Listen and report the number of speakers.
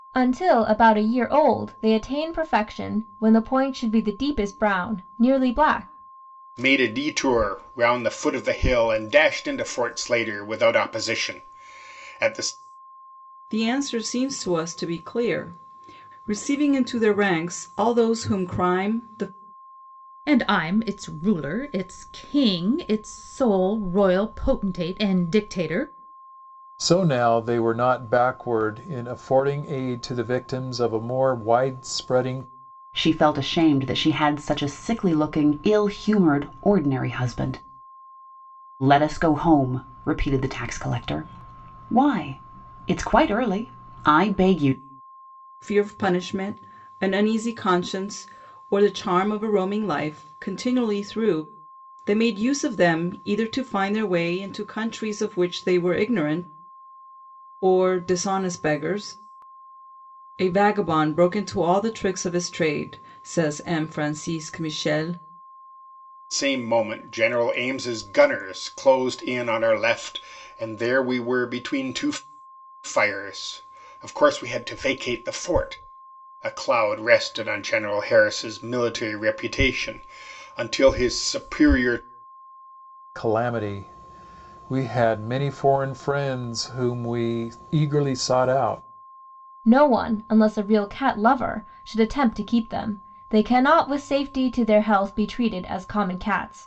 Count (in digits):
6